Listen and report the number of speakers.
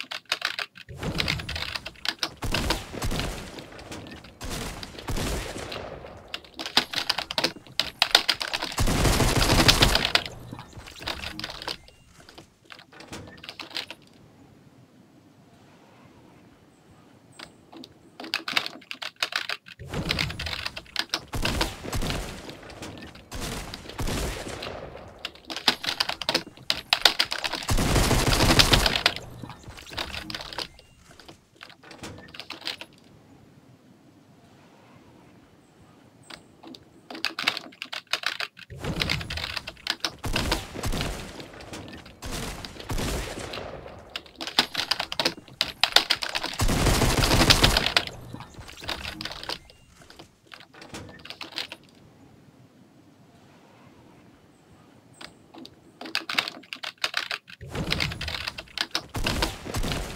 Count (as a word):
zero